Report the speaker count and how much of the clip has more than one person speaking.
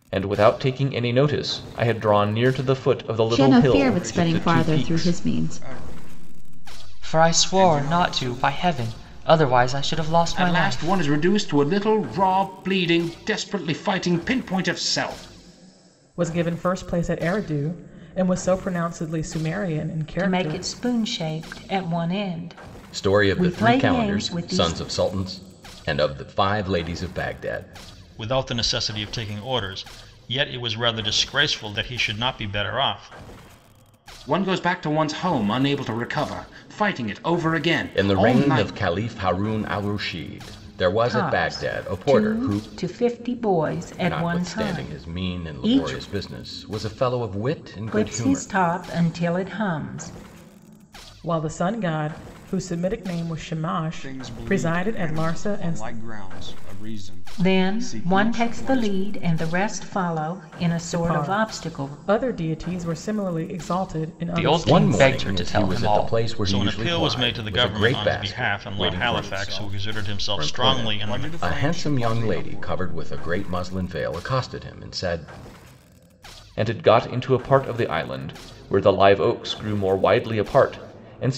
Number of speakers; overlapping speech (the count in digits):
9, about 31%